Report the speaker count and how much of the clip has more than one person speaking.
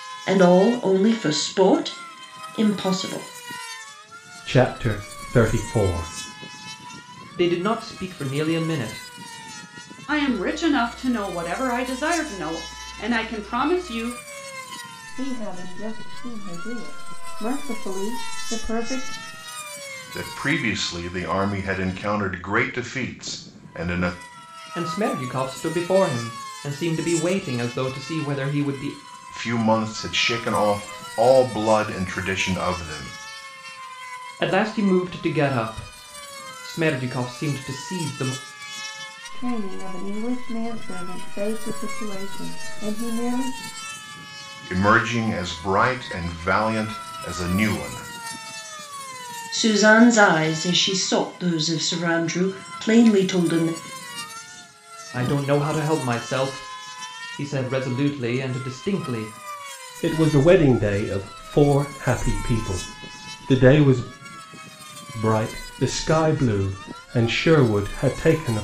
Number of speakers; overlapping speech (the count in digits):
6, no overlap